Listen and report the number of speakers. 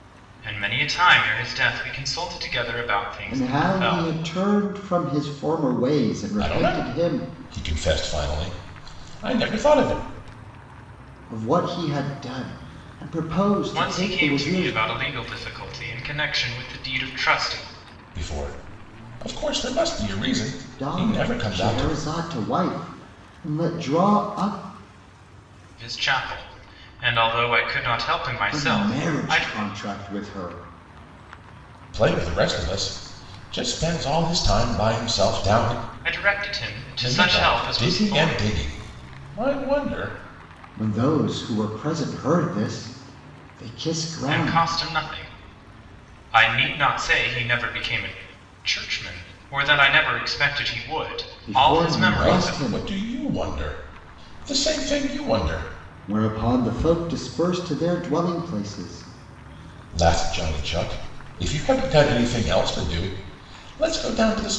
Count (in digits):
3